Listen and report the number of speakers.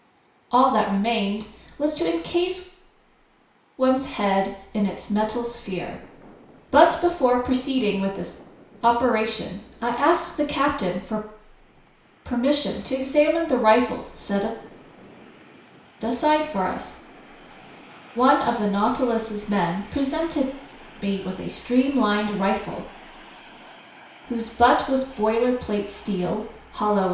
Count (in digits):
1